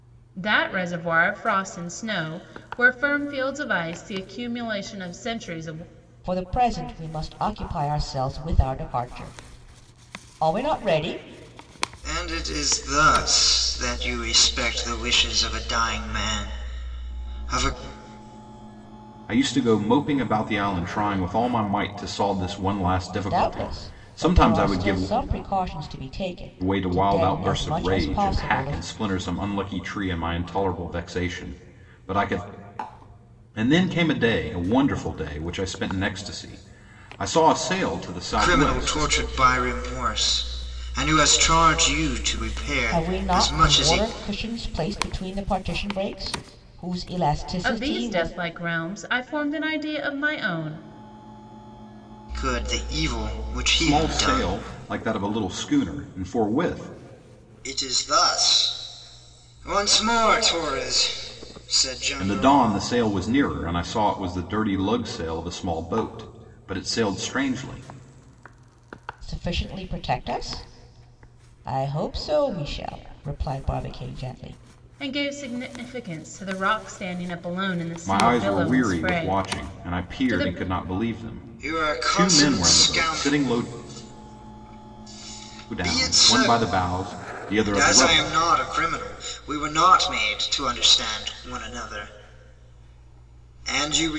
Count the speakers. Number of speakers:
four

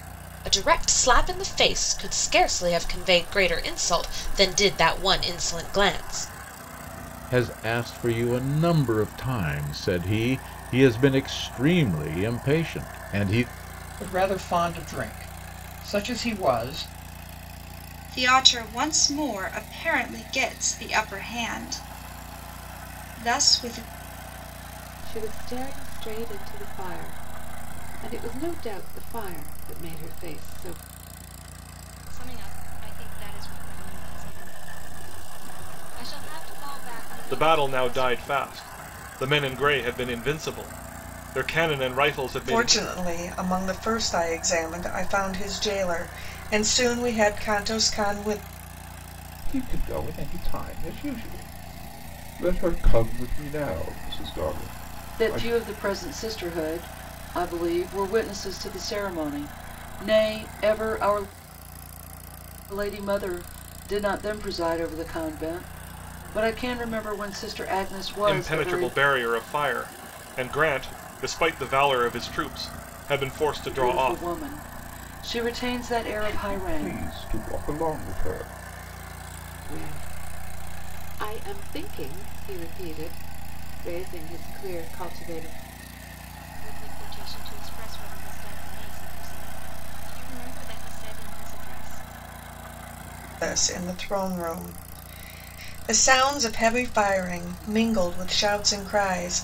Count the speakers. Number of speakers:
ten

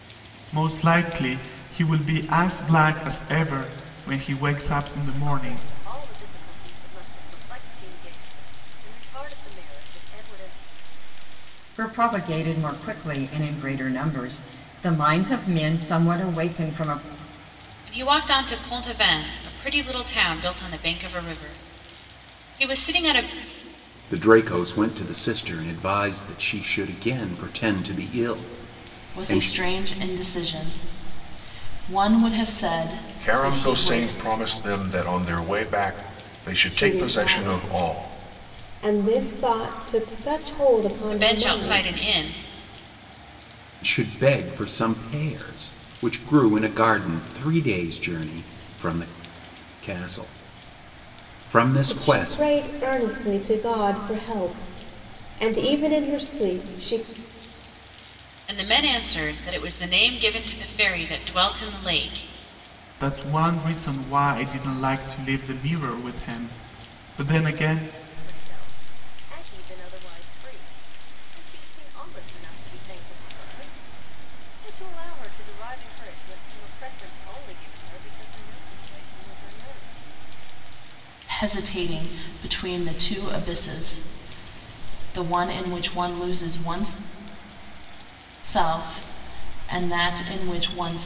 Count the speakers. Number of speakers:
eight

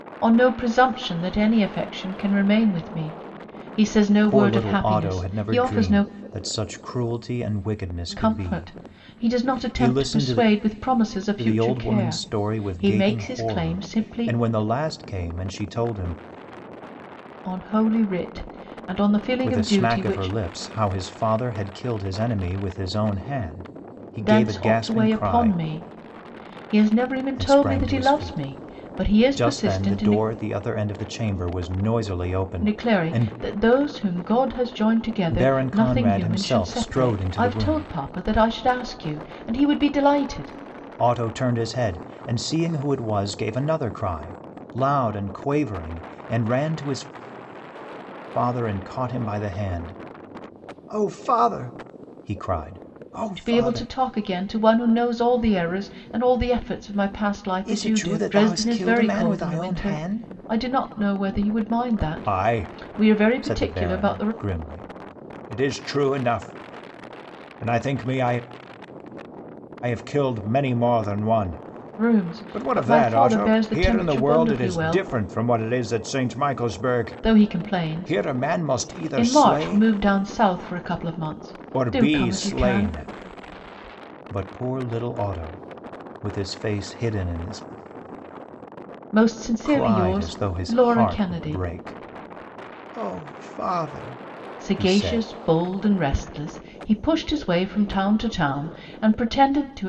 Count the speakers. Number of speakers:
two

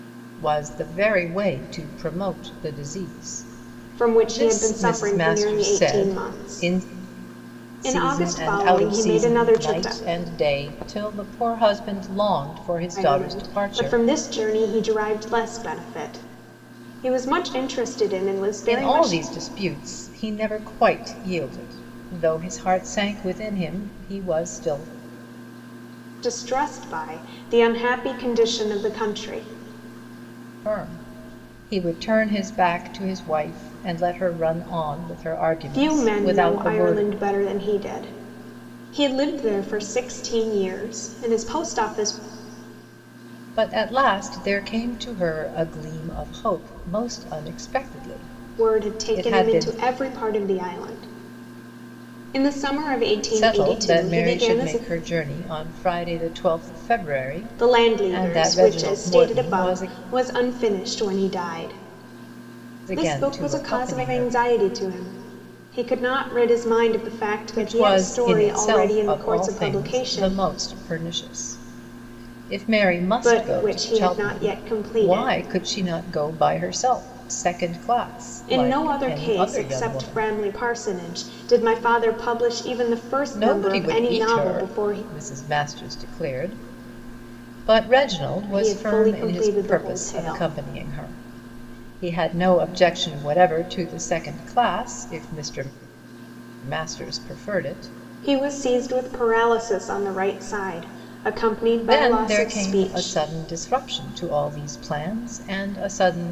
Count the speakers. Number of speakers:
two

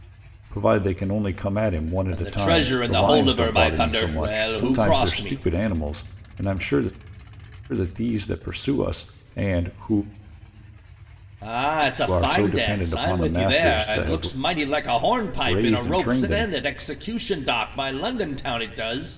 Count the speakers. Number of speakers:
two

